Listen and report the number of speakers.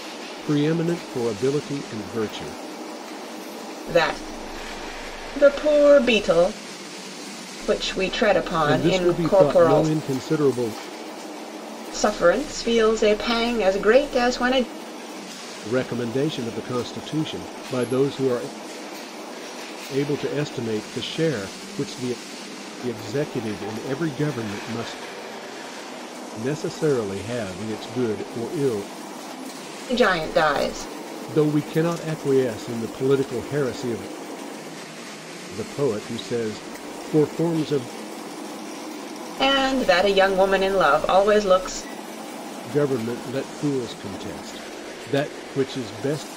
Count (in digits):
2